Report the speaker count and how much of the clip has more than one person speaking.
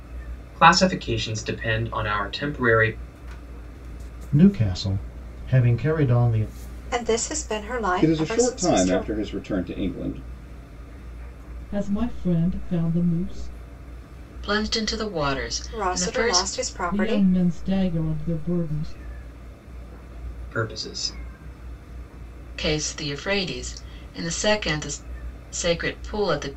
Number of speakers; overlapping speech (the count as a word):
six, about 9%